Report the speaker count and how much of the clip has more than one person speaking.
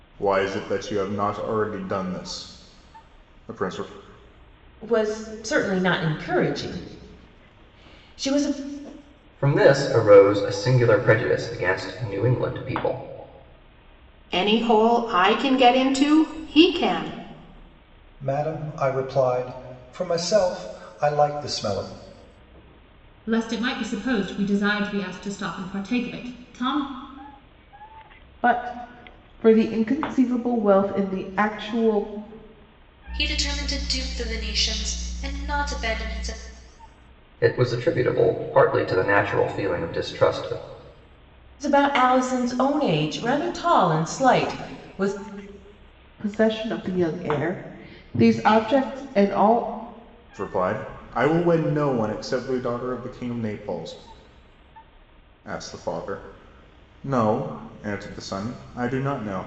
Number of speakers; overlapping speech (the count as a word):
eight, no overlap